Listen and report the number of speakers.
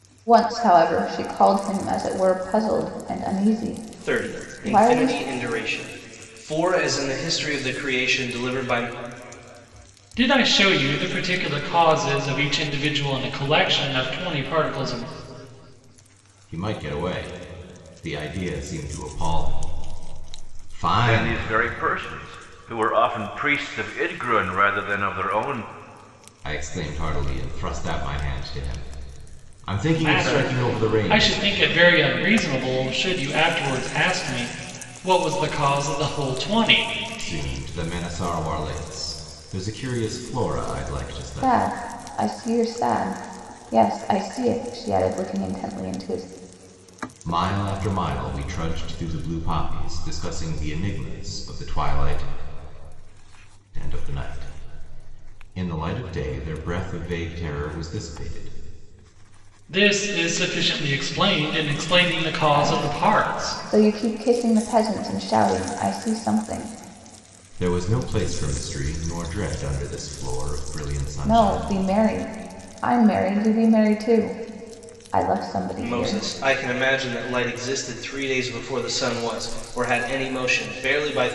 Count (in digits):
5